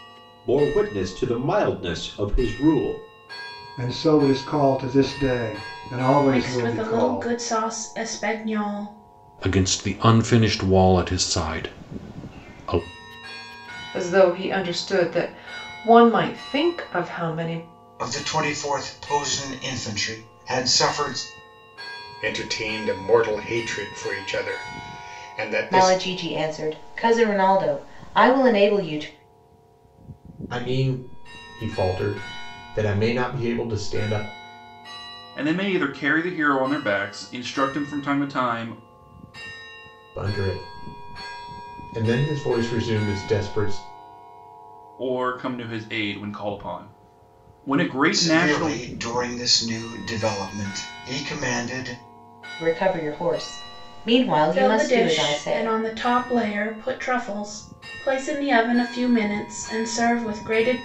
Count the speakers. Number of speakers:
10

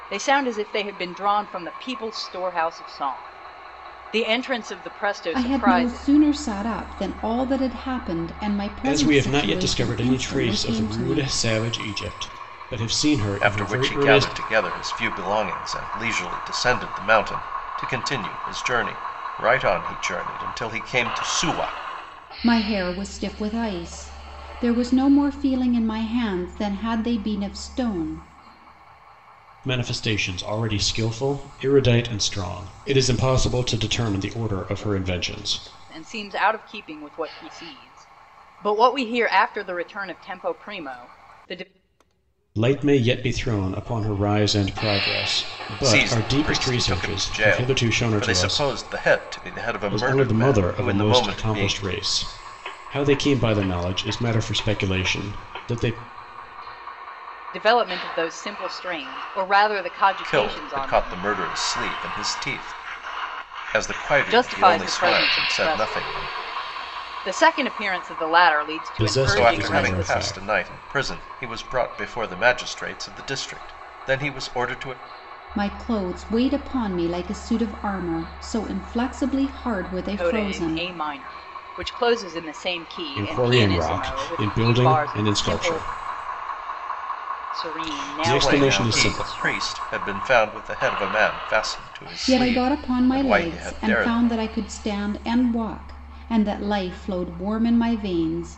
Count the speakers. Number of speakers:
4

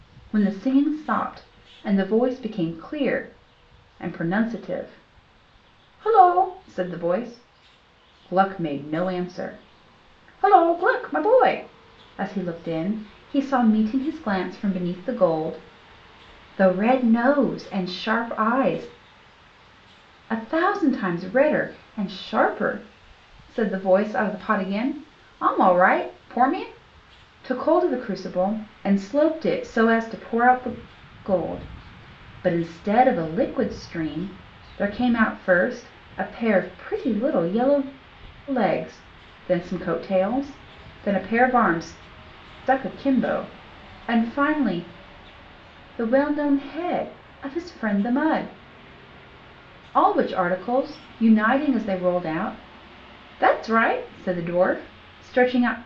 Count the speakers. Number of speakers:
1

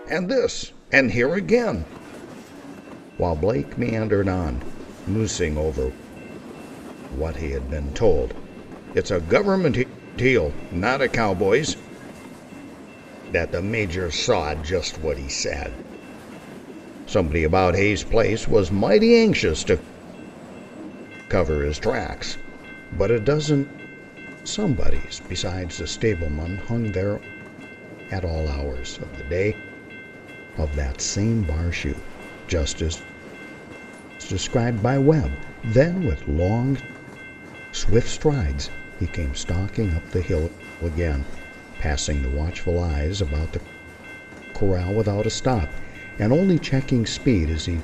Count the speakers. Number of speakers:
1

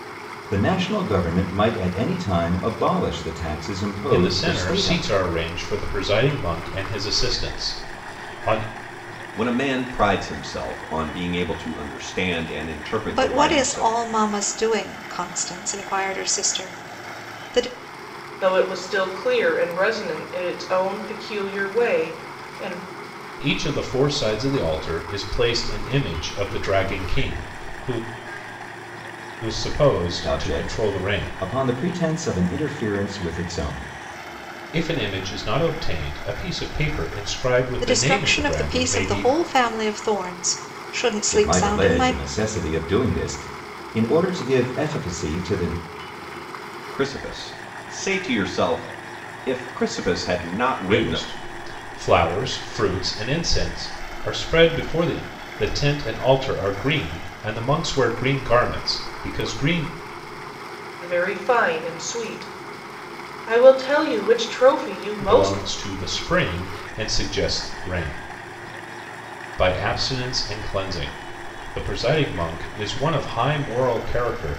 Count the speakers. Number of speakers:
5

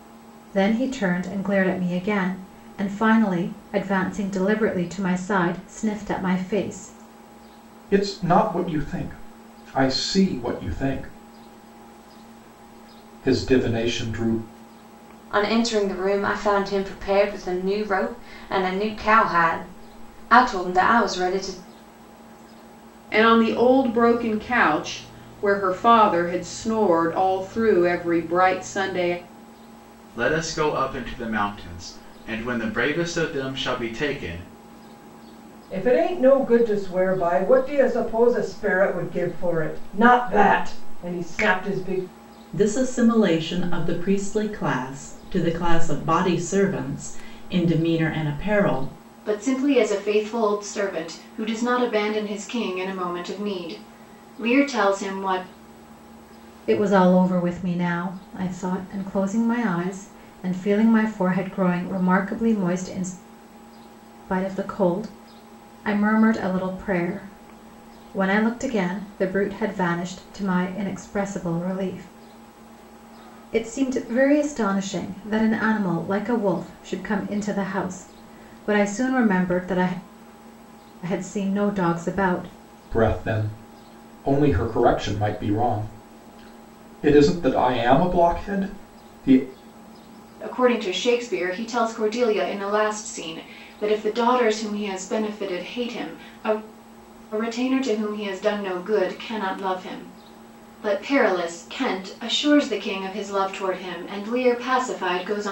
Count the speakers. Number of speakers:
8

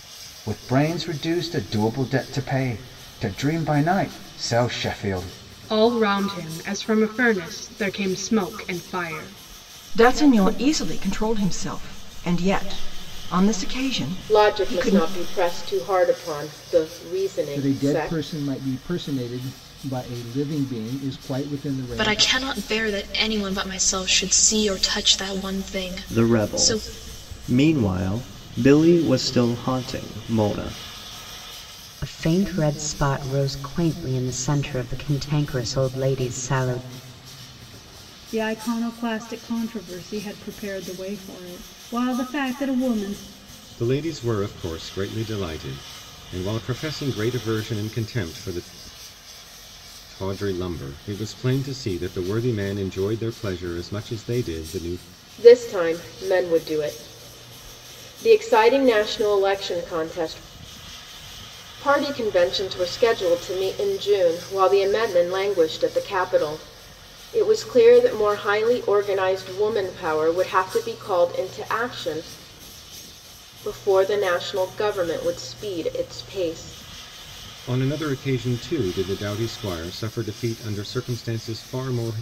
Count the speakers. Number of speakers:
10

